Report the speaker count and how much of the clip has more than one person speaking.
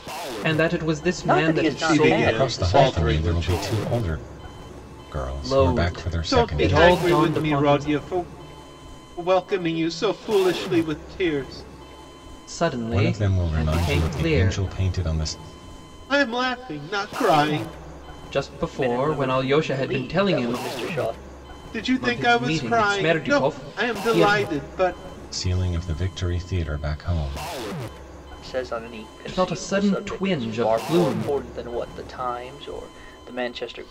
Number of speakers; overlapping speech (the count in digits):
4, about 38%